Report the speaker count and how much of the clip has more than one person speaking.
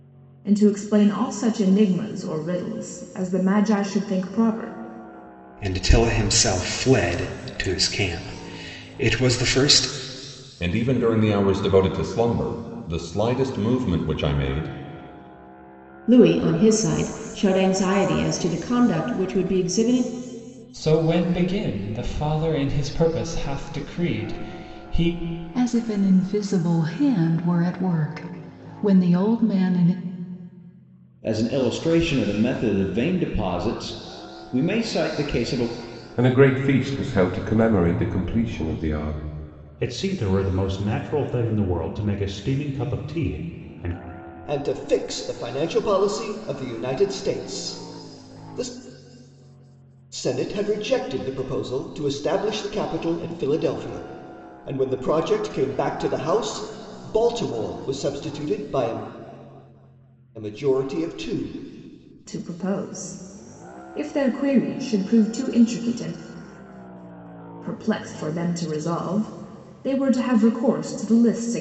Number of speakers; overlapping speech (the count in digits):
10, no overlap